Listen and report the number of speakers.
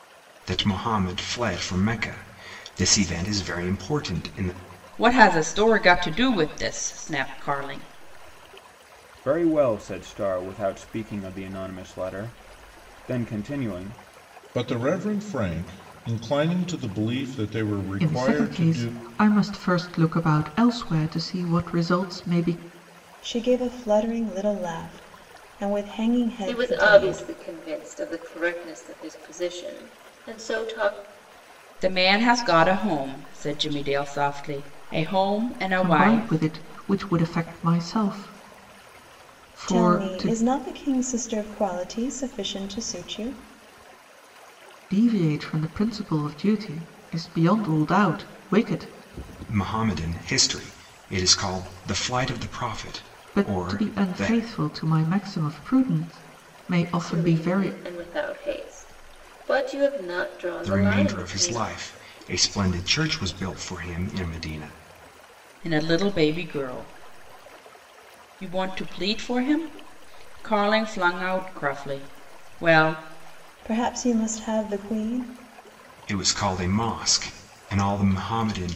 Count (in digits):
7